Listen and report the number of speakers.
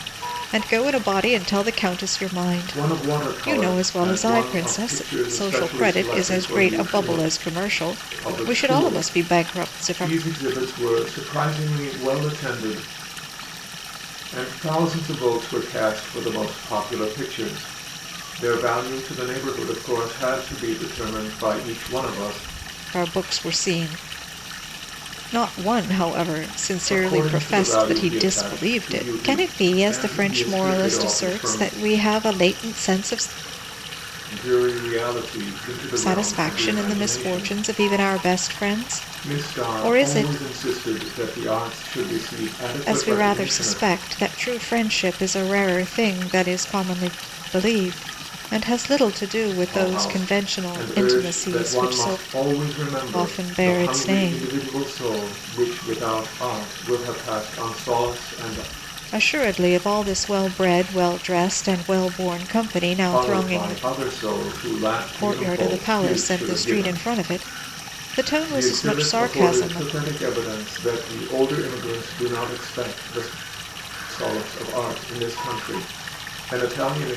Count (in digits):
2